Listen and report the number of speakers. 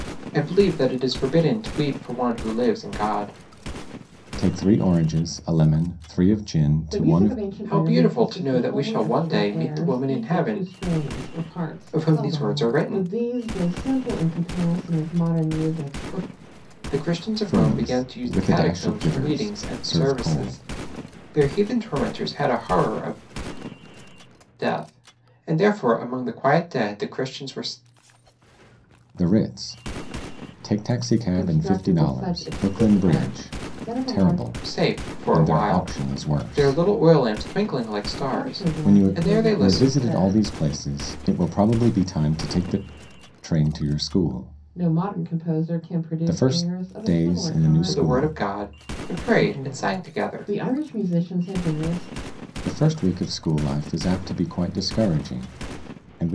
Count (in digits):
3